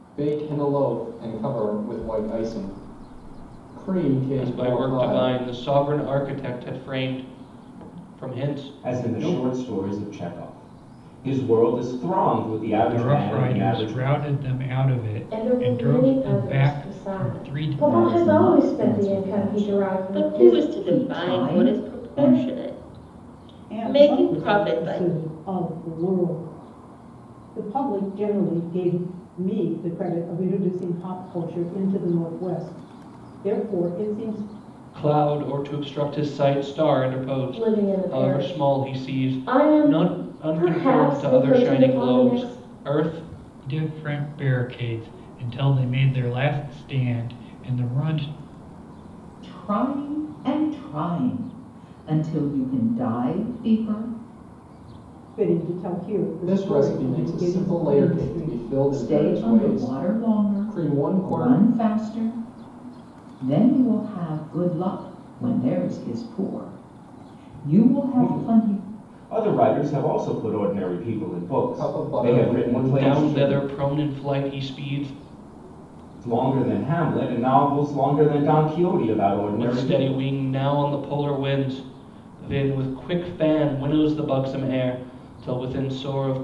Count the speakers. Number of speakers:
eight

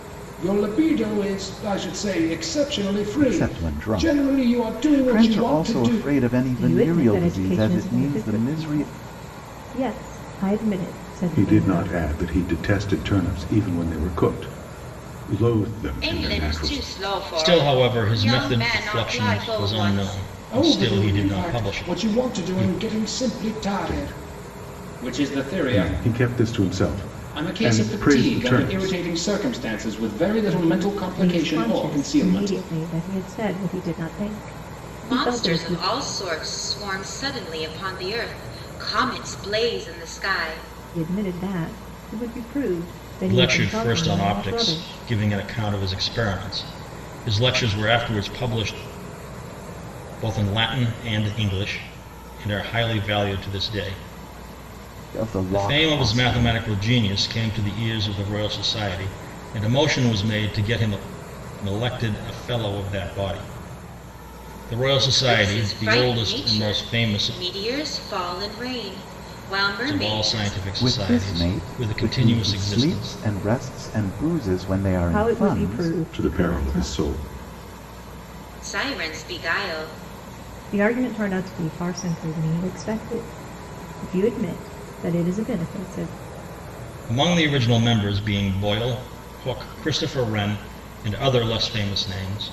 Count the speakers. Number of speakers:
six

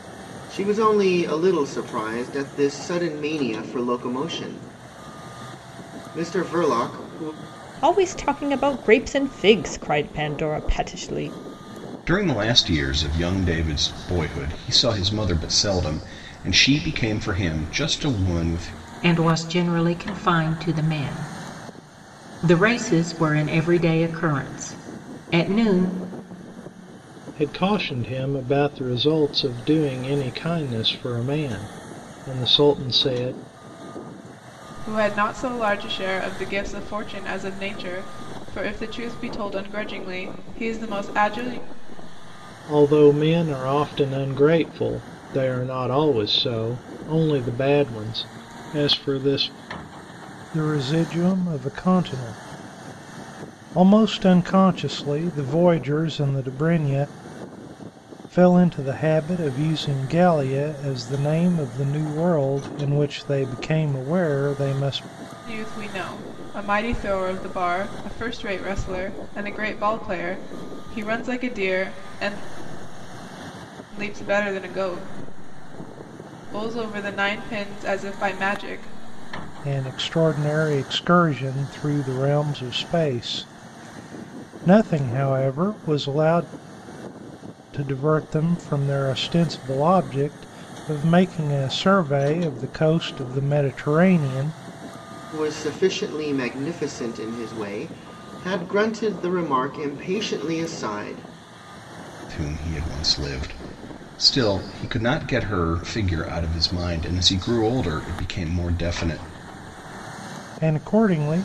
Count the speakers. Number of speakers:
six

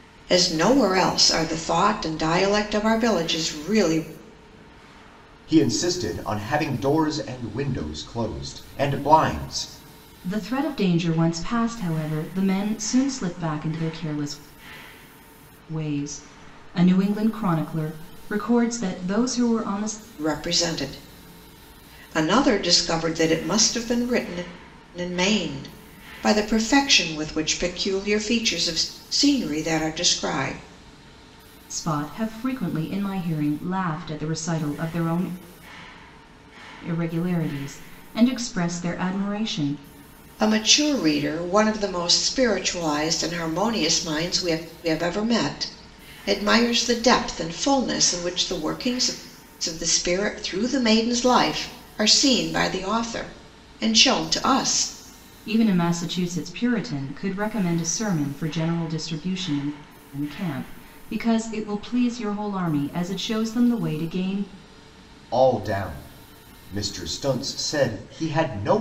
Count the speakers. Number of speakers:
three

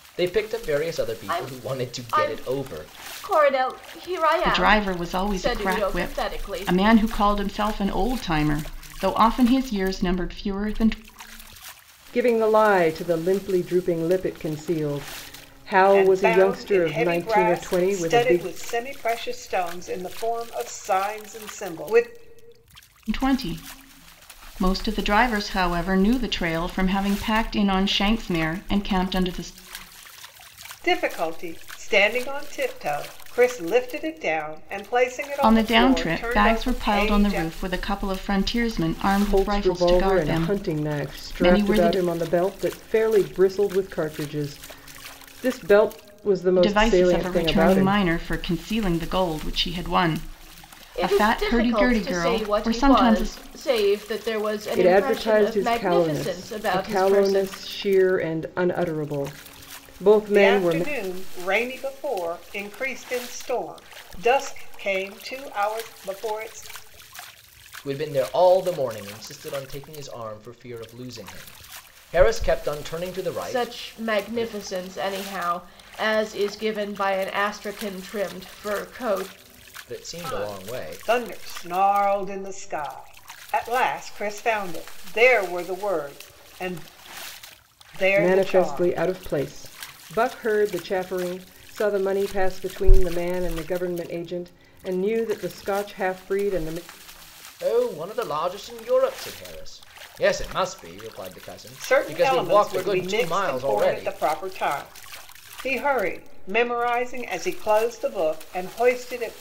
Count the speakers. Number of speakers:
five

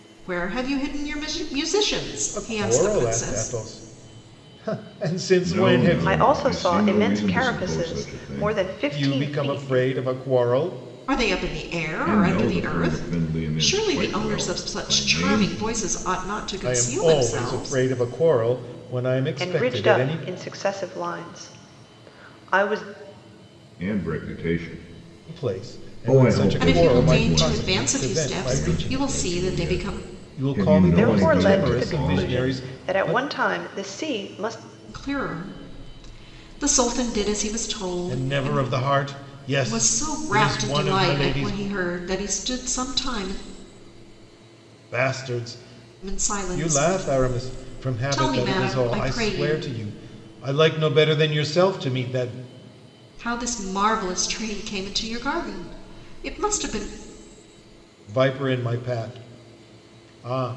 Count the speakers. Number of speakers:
four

